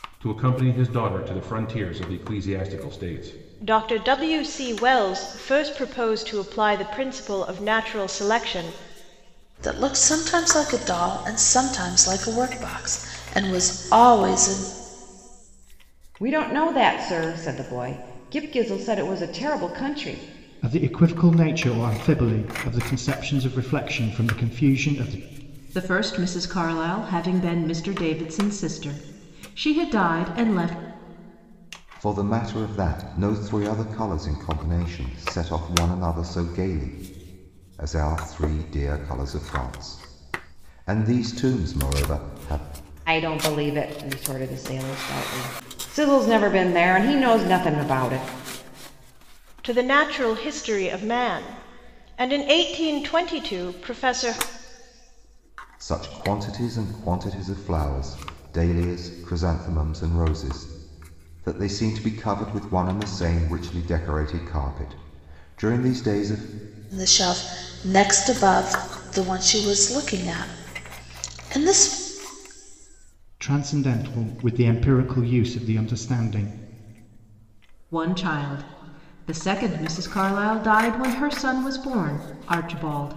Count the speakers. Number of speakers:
seven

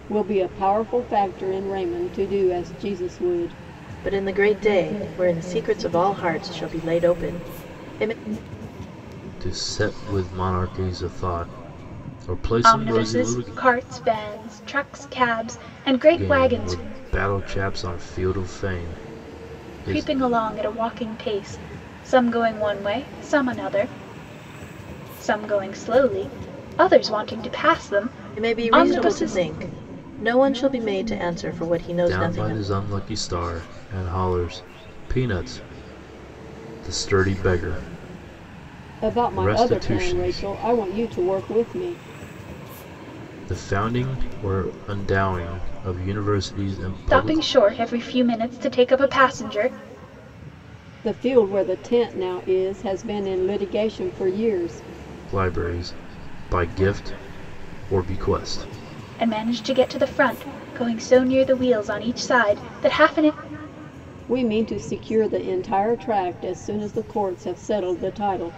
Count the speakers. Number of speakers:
four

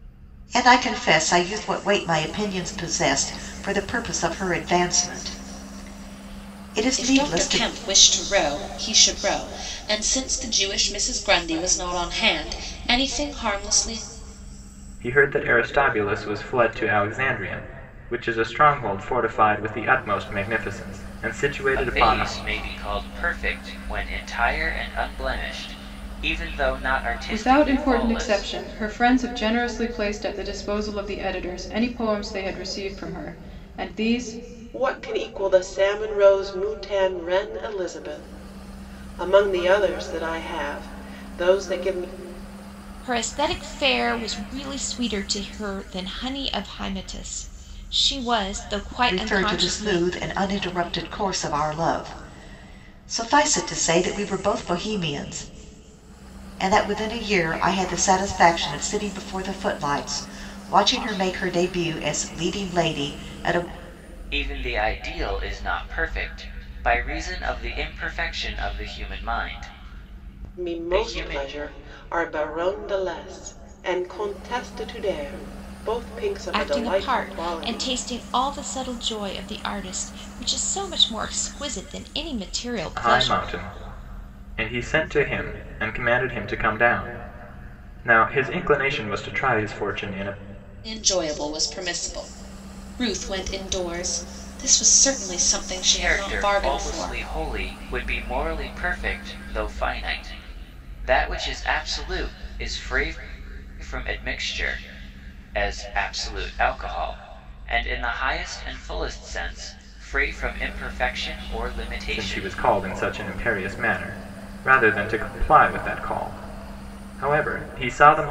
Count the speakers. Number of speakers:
seven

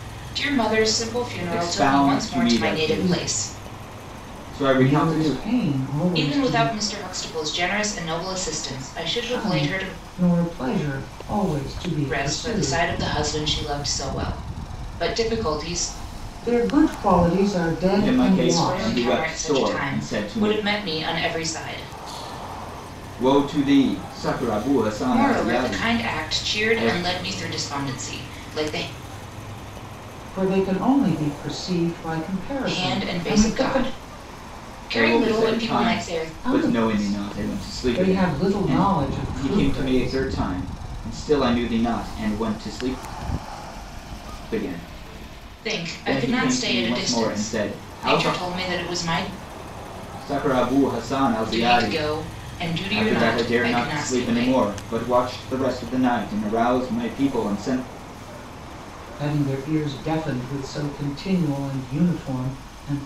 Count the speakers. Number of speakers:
three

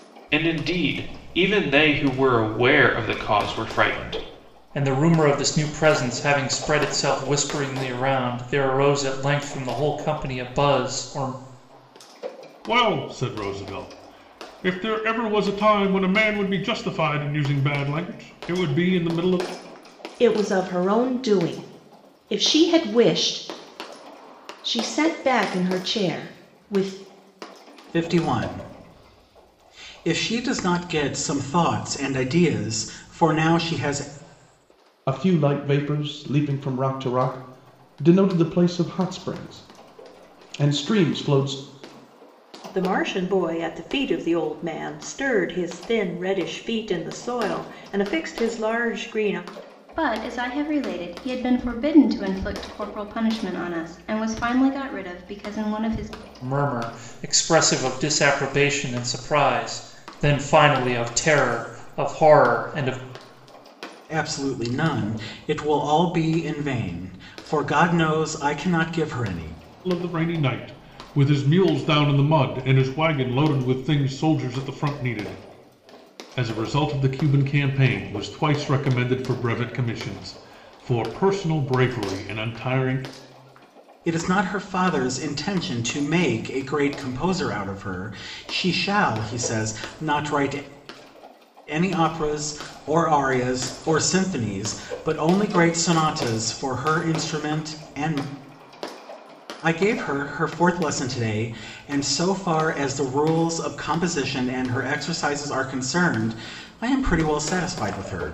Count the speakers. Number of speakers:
eight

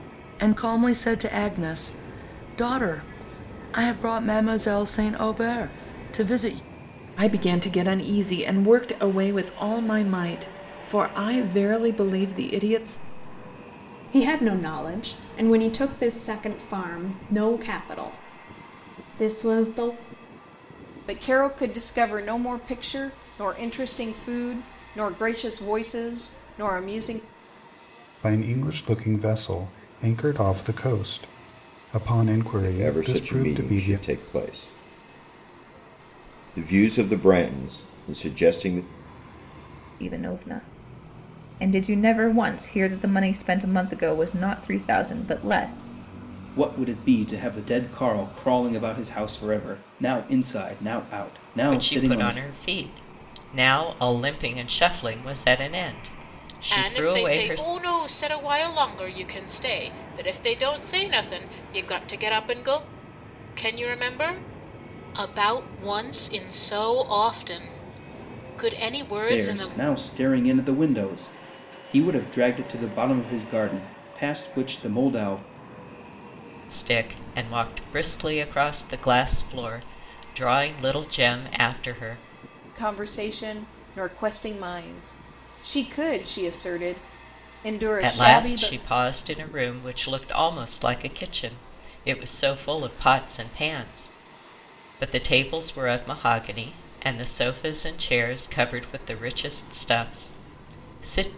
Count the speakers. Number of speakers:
ten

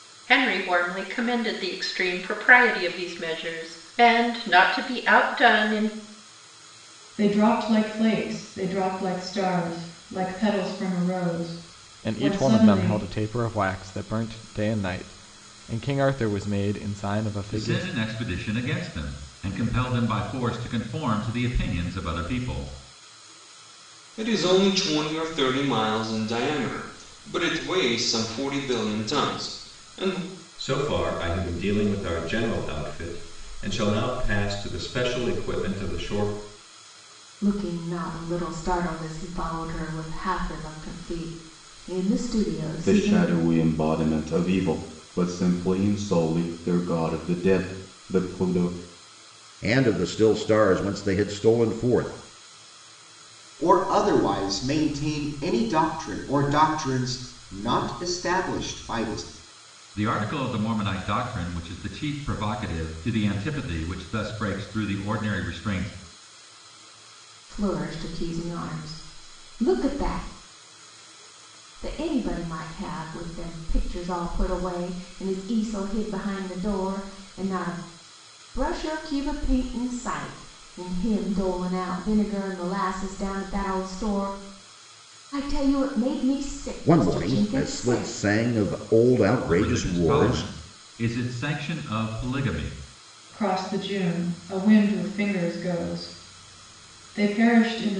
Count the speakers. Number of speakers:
ten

